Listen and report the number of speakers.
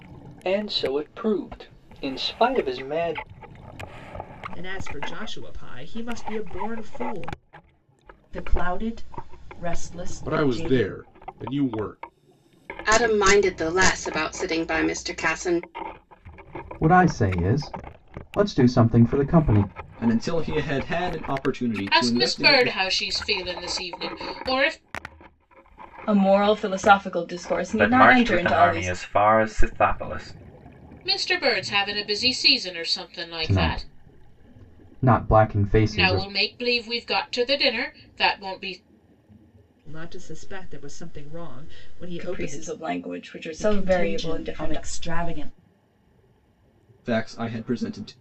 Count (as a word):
ten